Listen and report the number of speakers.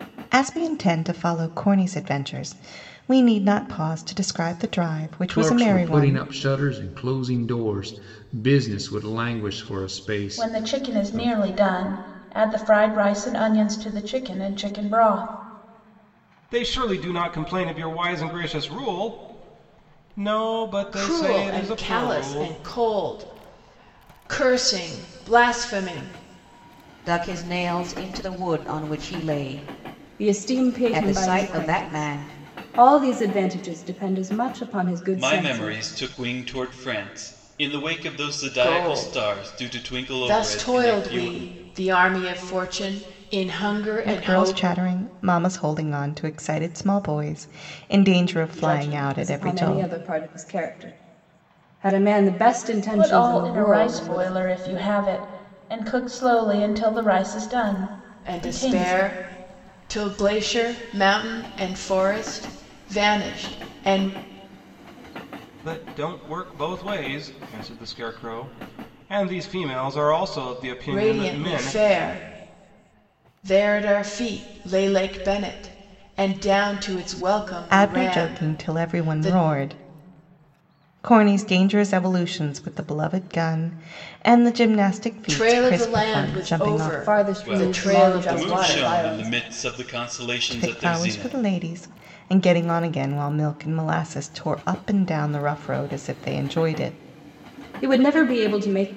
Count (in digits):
8